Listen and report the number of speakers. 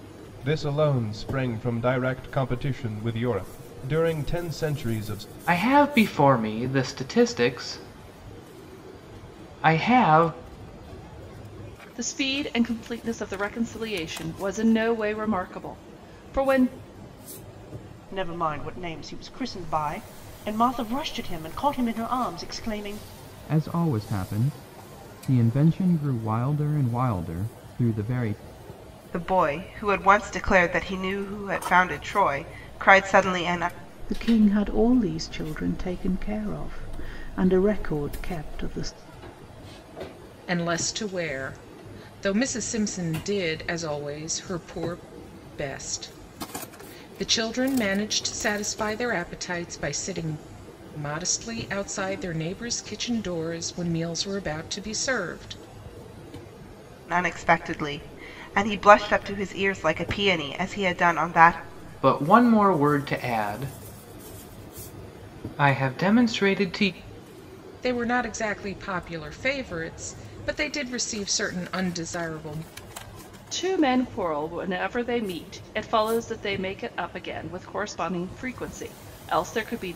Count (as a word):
eight